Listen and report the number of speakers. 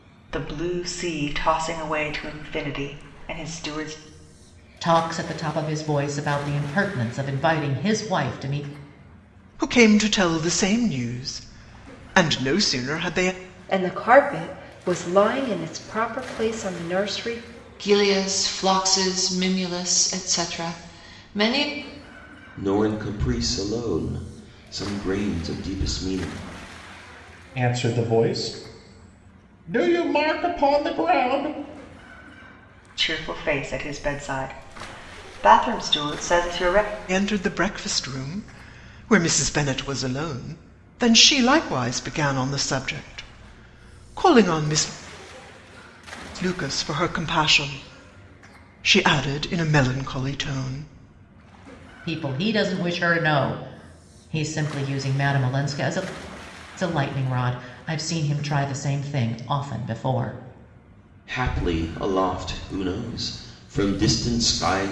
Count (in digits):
7